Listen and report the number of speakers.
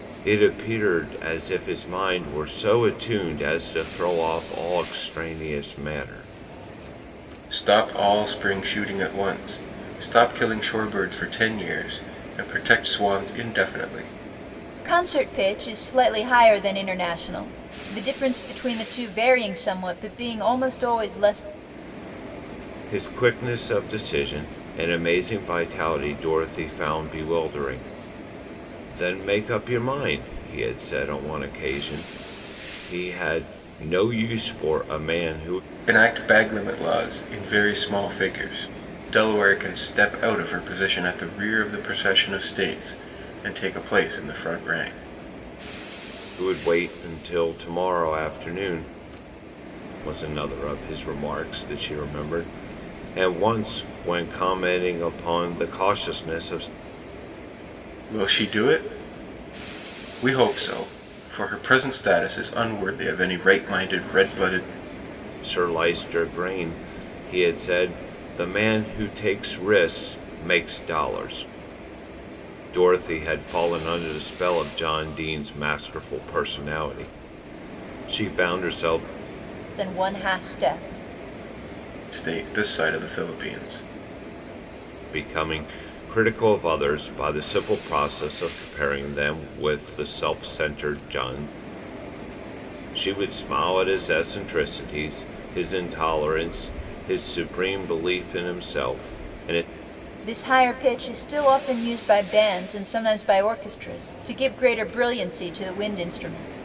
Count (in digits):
3